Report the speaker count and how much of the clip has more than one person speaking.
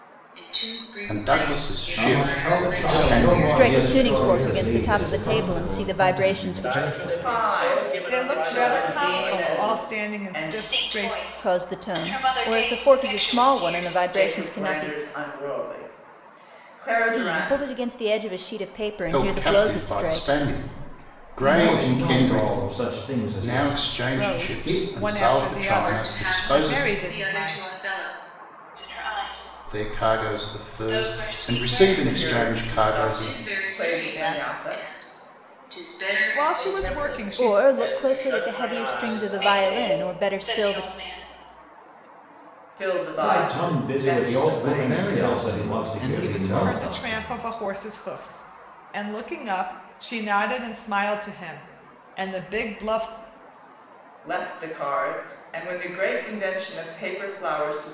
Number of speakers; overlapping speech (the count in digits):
10, about 63%